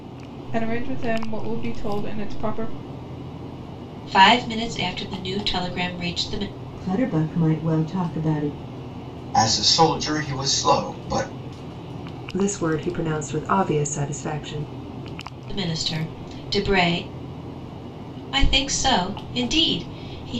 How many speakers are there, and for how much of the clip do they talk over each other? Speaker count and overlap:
5, no overlap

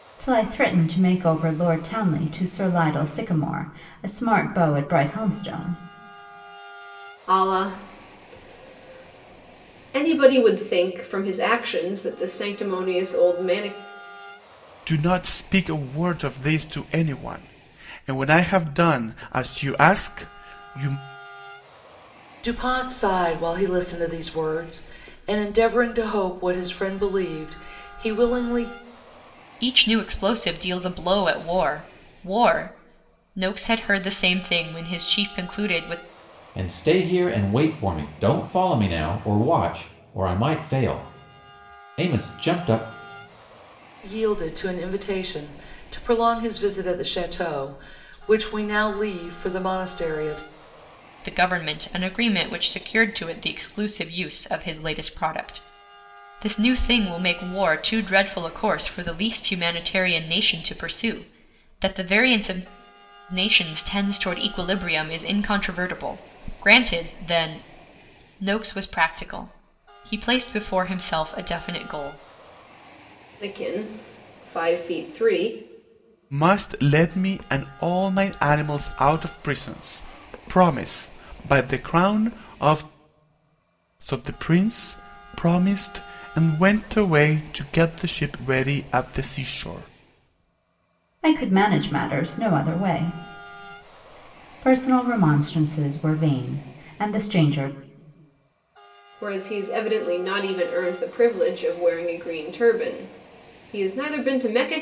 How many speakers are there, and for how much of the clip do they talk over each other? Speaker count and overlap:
6, no overlap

